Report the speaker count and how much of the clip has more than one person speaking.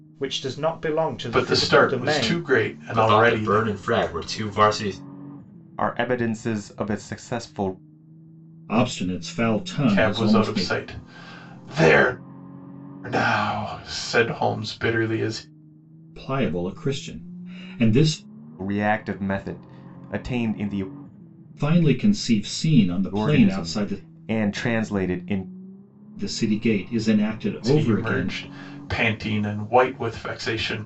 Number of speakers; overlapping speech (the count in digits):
5, about 15%